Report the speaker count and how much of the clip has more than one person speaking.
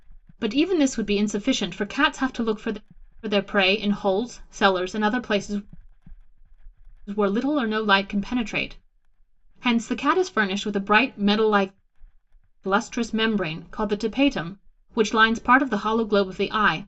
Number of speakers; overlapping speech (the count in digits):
1, no overlap